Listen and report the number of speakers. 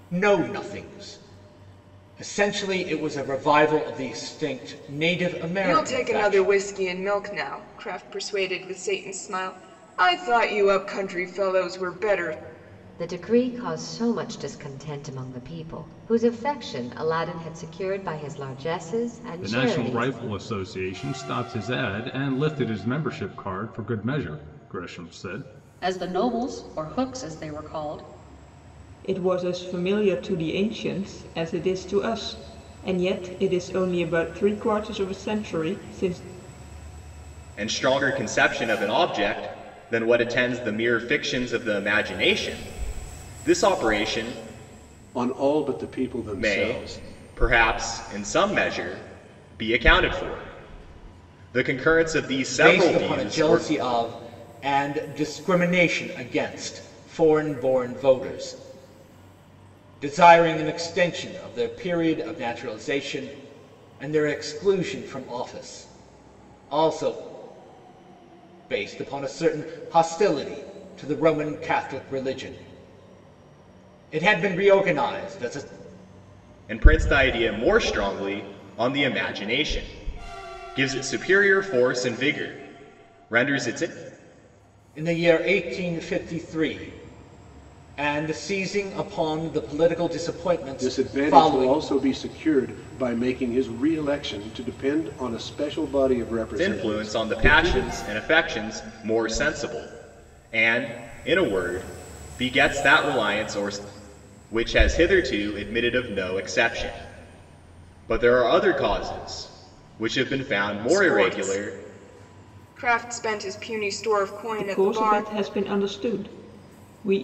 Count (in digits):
8